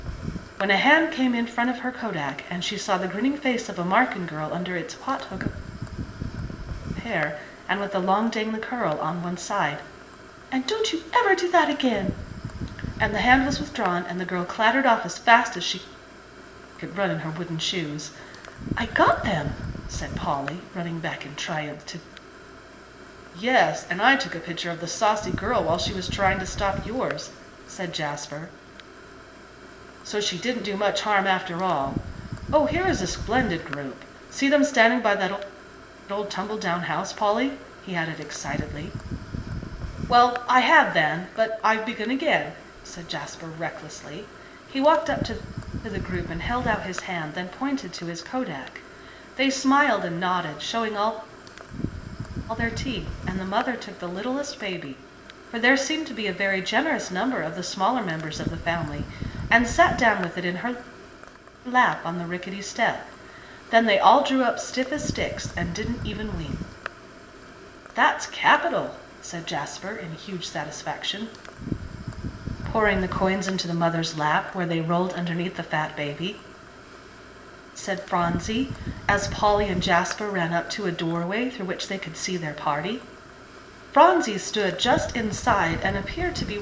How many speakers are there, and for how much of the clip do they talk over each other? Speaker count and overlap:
1, no overlap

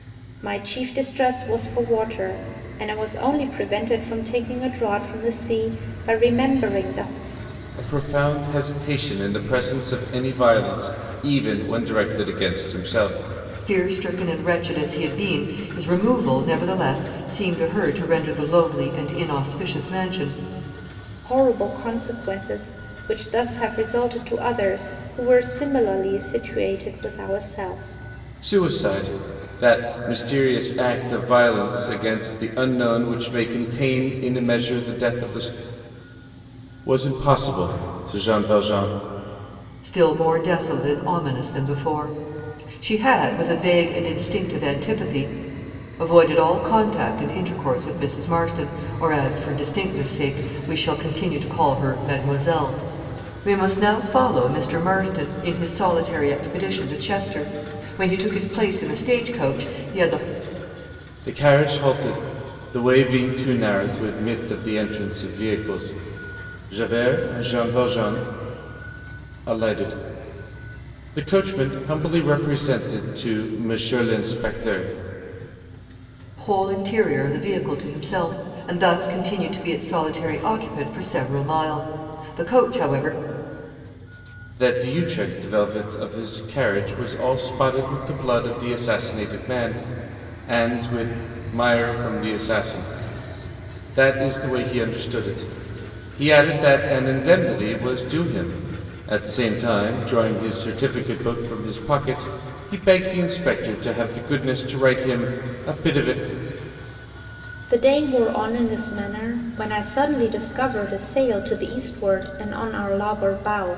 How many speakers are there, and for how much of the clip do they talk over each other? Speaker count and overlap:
3, no overlap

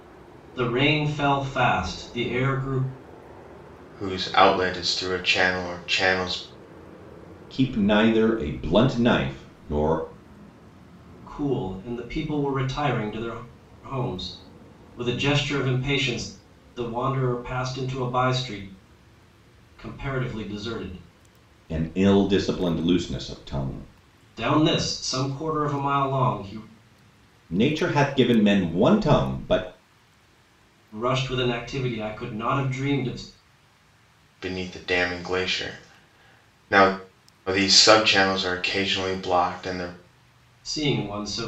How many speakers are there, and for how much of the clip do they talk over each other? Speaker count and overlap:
3, no overlap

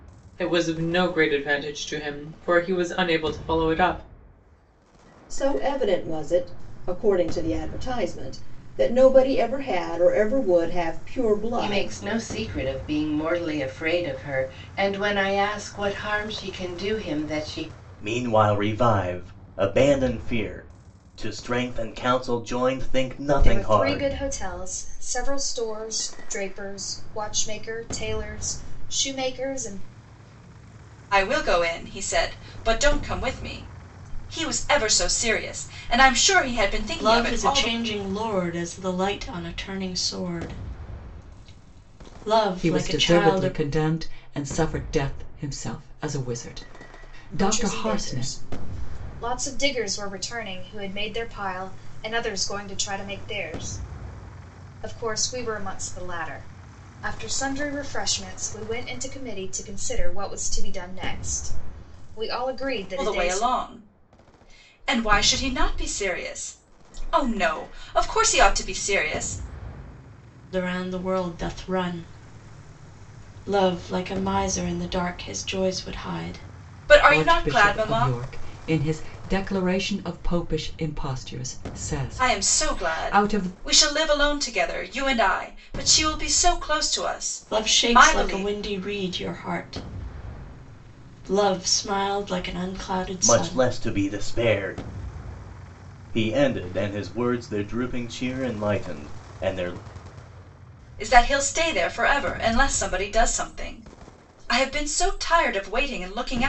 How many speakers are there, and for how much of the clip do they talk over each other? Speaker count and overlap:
8, about 8%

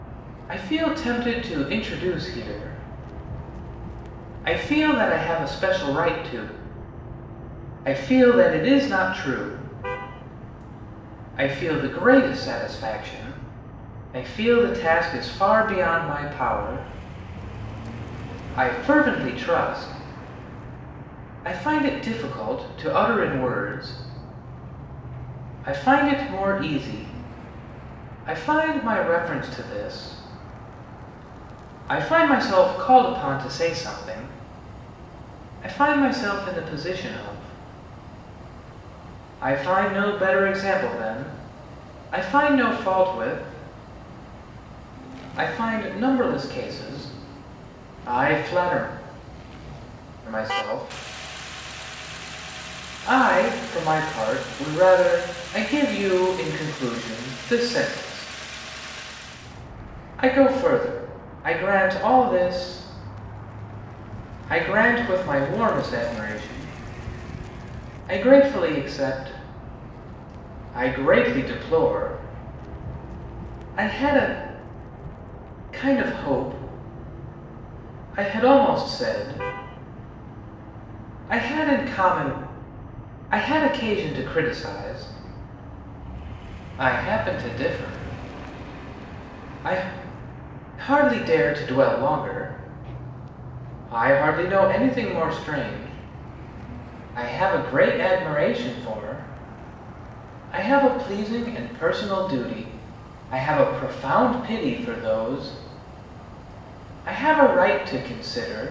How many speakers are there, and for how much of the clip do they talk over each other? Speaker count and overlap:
1, no overlap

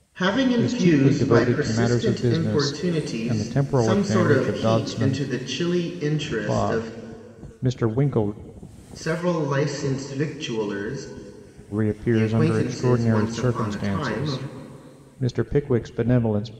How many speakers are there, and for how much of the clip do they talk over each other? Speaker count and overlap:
2, about 44%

